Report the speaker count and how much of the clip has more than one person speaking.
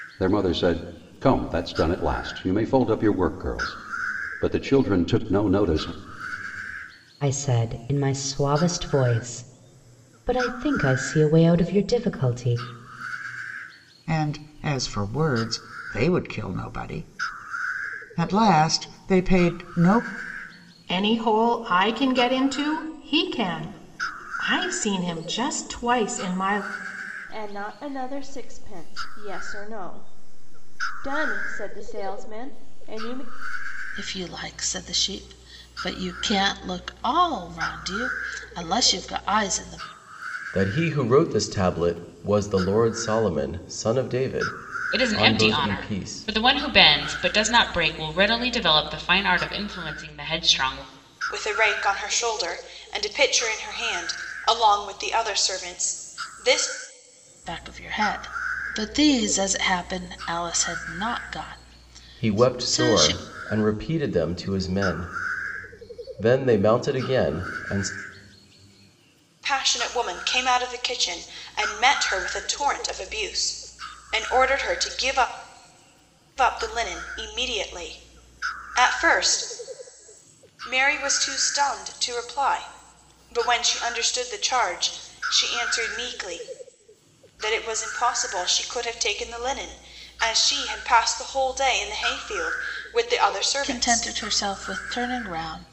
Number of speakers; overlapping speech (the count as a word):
nine, about 3%